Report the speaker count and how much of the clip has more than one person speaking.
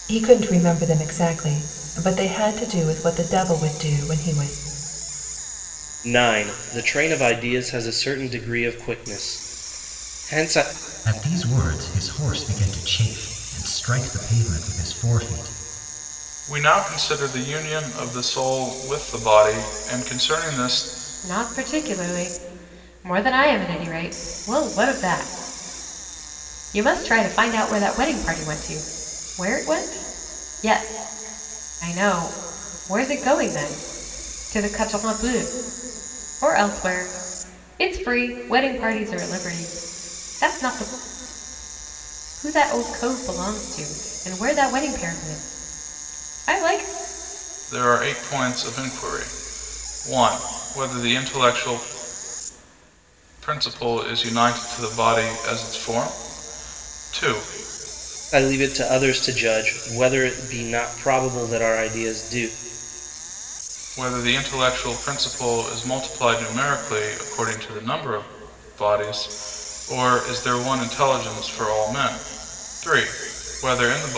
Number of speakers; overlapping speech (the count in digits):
5, no overlap